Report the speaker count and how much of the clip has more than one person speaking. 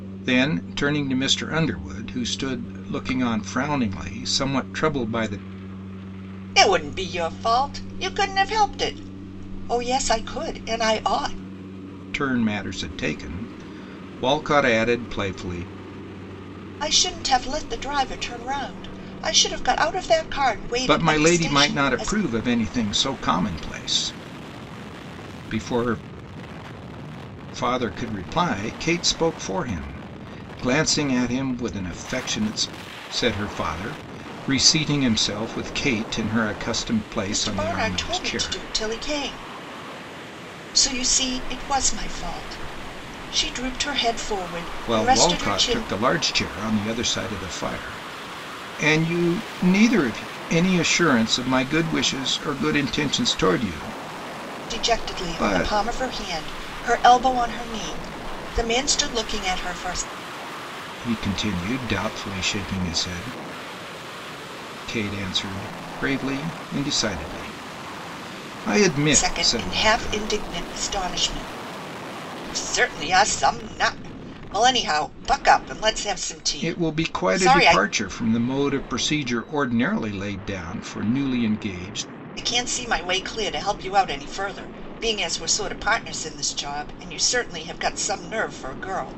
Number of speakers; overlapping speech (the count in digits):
2, about 8%